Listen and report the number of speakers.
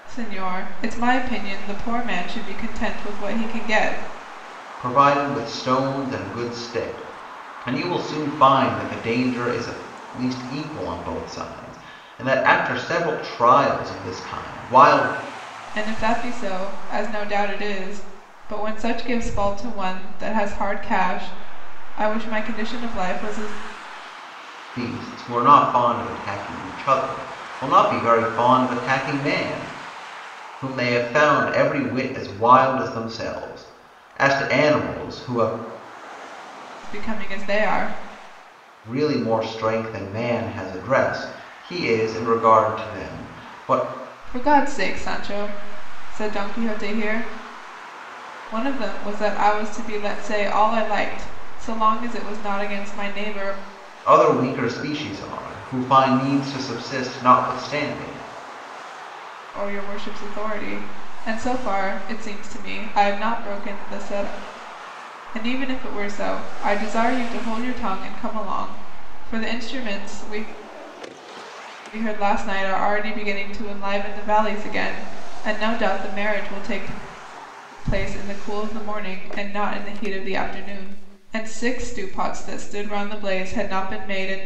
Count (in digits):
2